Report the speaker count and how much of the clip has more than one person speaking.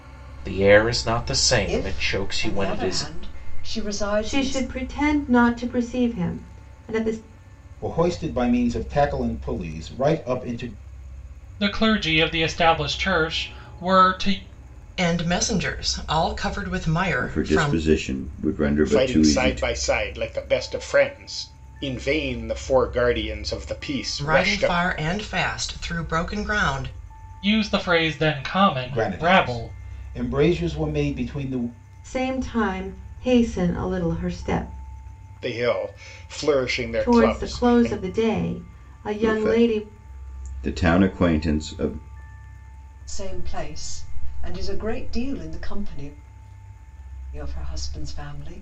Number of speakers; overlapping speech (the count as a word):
eight, about 14%